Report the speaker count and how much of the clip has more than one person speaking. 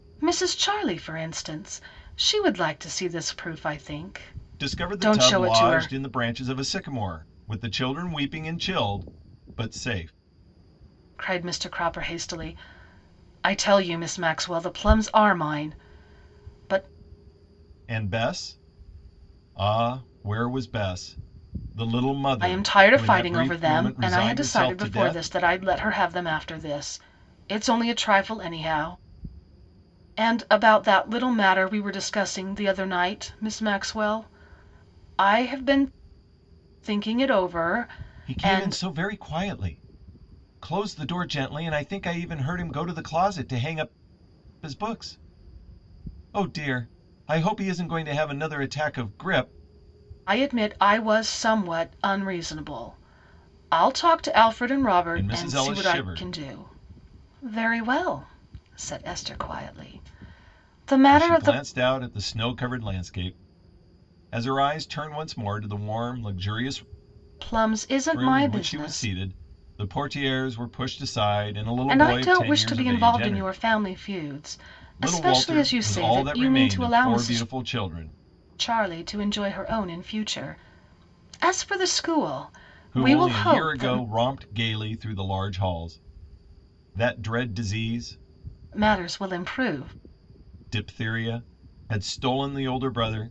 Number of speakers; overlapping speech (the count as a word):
two, about 14%